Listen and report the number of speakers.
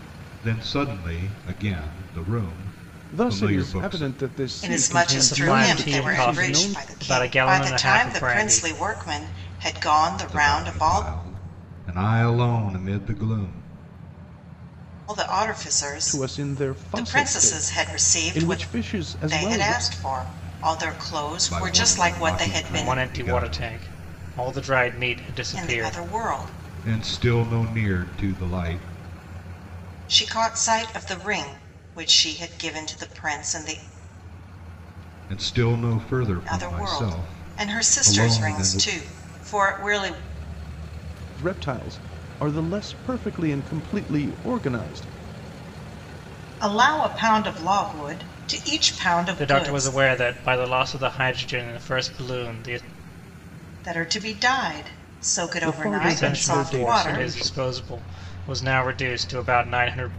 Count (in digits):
4